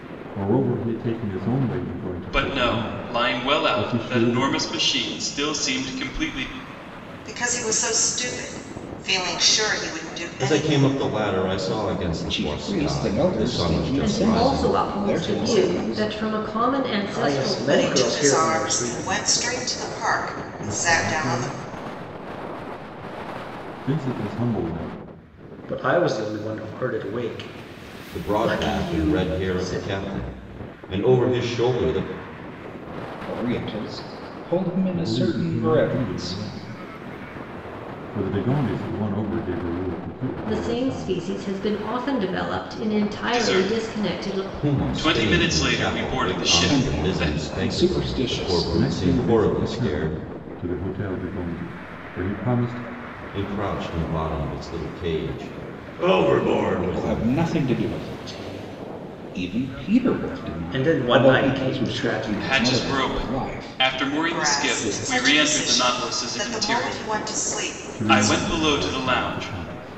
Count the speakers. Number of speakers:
seven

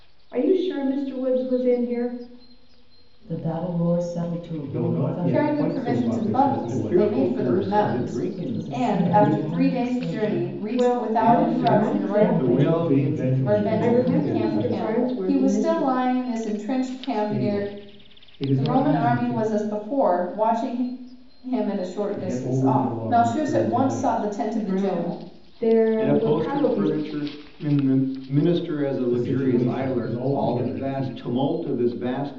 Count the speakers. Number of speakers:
five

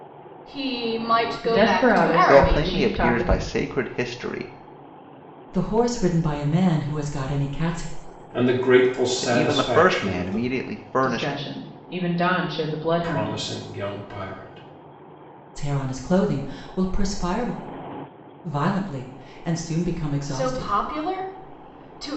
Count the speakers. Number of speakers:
five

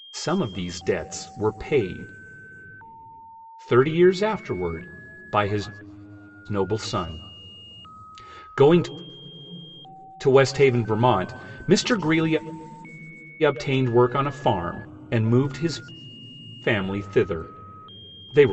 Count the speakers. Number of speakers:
one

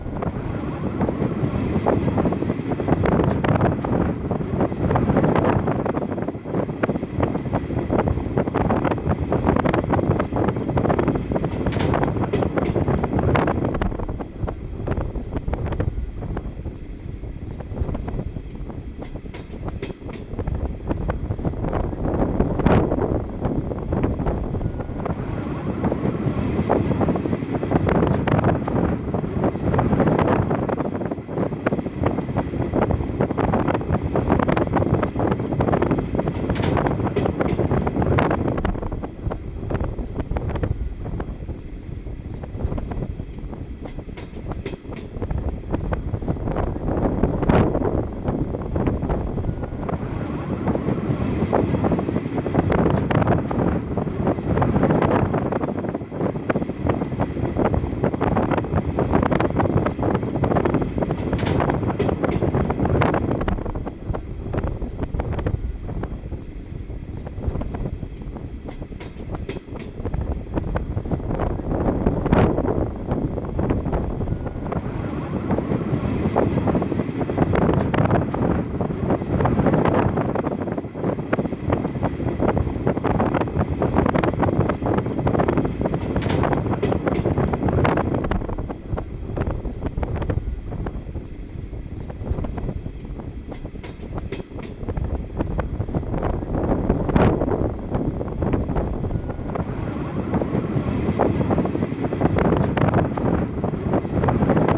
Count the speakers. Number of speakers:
zero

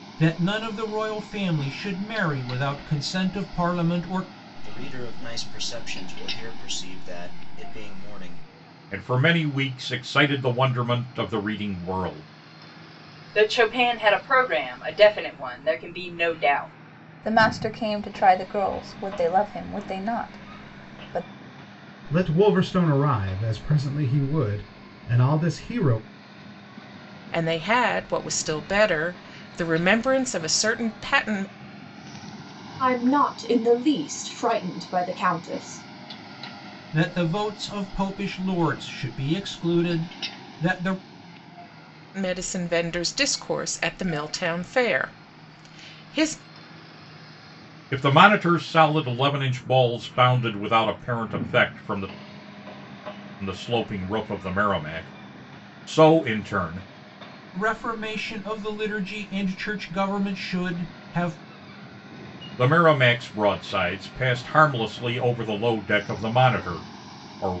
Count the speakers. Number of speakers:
eight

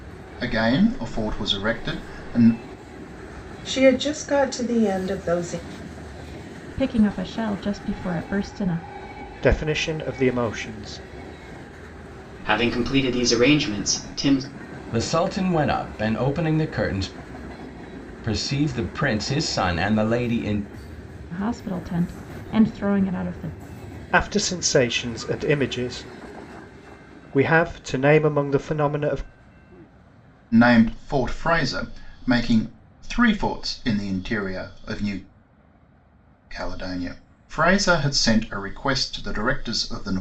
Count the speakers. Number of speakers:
six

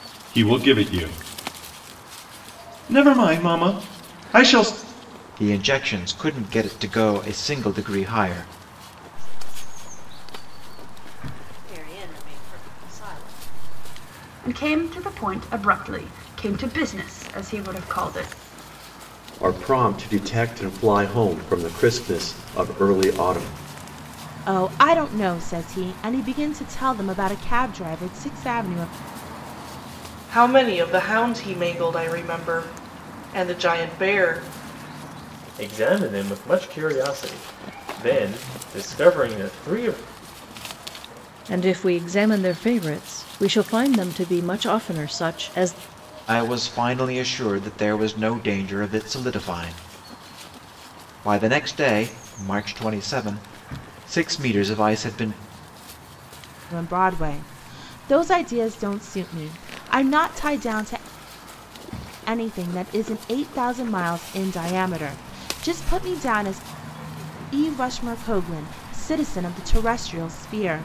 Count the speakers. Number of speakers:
nine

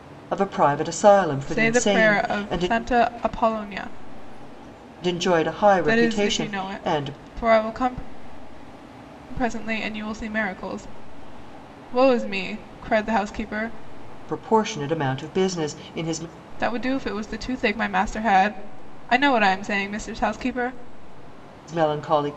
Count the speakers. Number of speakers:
two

